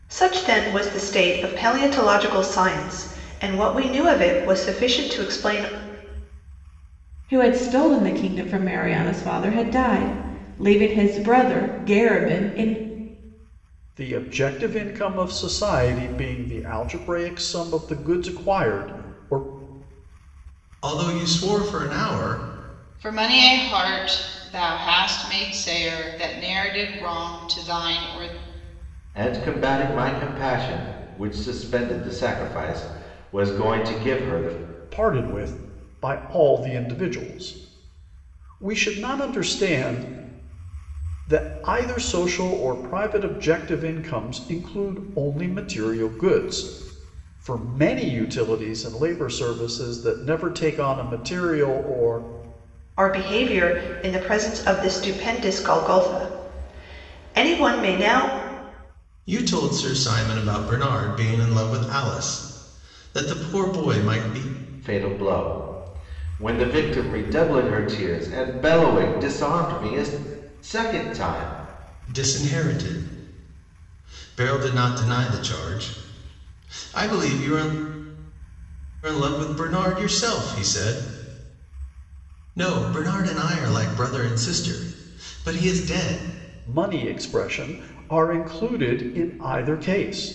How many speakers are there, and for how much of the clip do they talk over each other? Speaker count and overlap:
six, no overlap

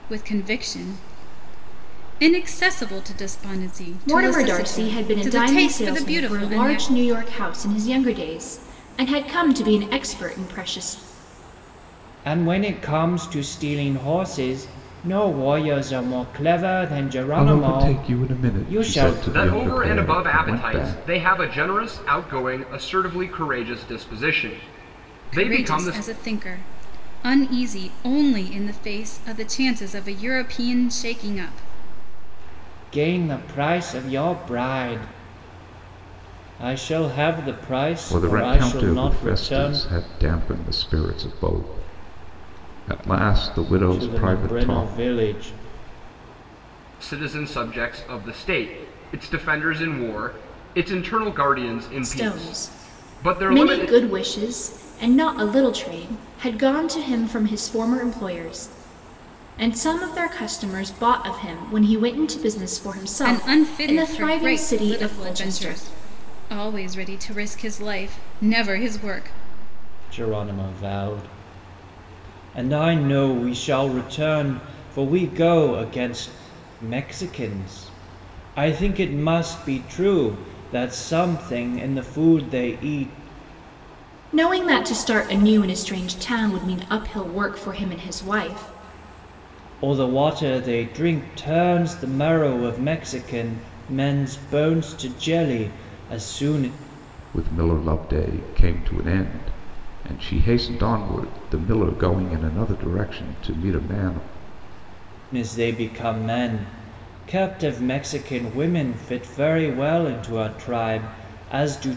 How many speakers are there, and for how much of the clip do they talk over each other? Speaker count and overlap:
five, about 13%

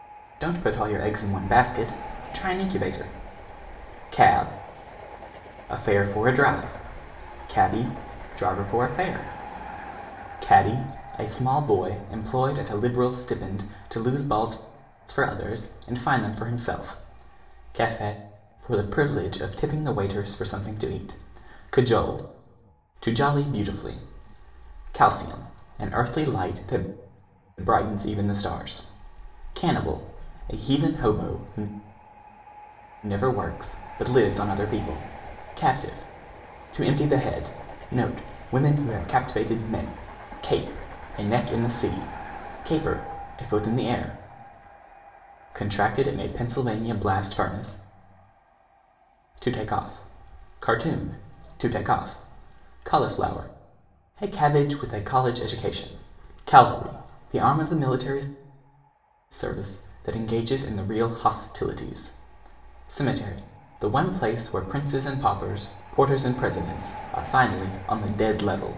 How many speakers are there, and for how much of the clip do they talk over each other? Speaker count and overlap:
one, no overlap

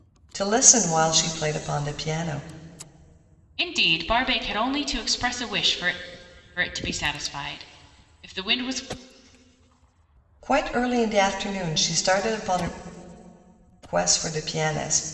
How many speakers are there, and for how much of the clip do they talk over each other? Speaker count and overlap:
two, no overlap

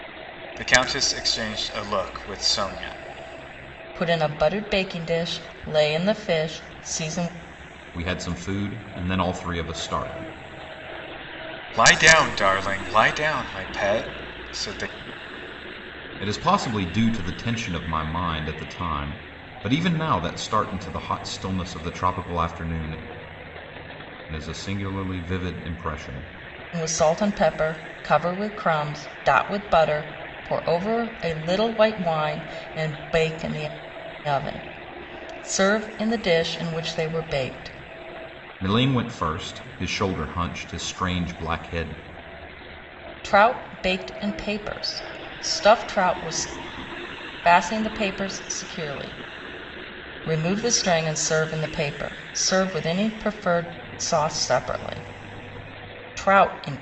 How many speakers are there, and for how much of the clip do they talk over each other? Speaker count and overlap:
three, no overlap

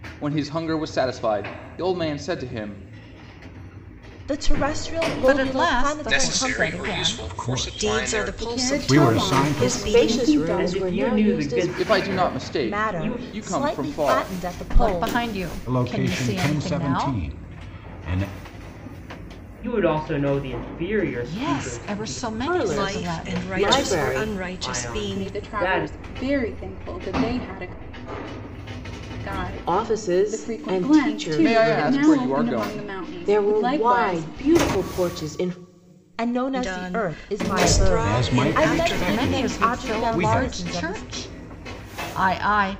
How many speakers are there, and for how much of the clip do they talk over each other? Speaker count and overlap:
nine, about 58%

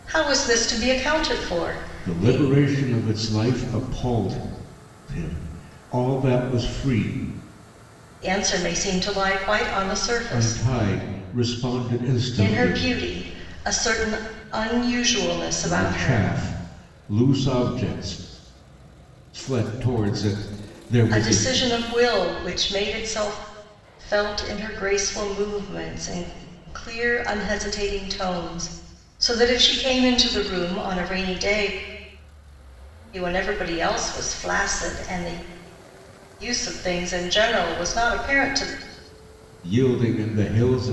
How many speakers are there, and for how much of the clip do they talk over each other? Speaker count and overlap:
two, about 5%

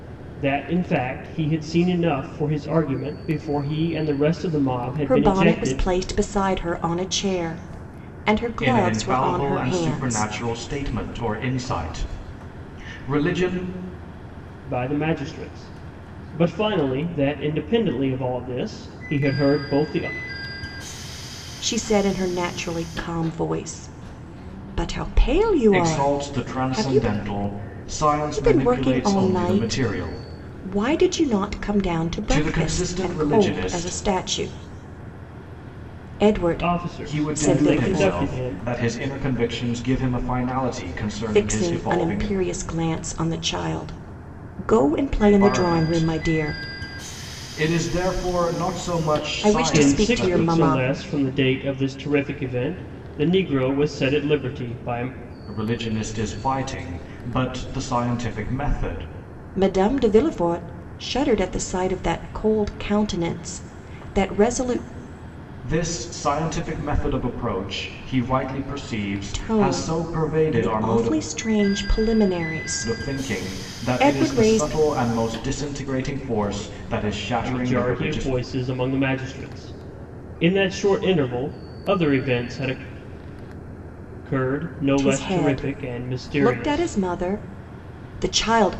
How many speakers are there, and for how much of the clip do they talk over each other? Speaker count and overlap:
three, about 23%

